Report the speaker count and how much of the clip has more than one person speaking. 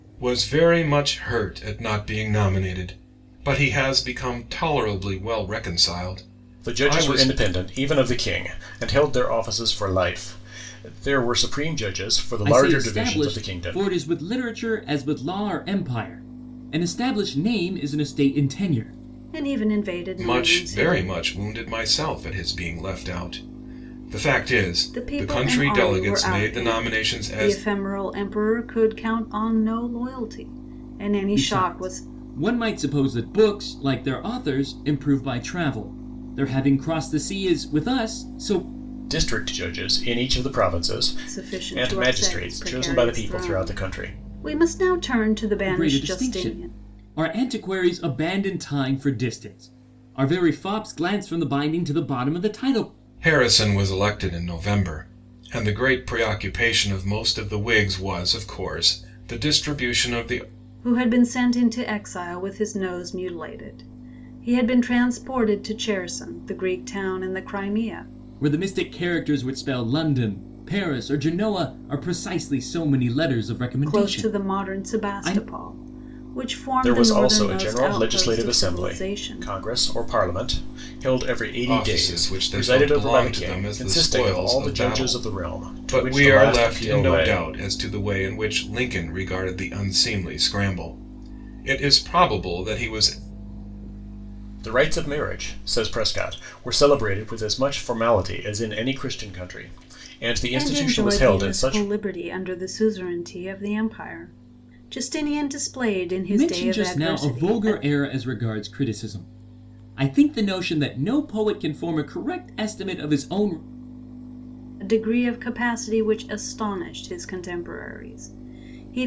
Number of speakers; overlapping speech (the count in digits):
4, about 19%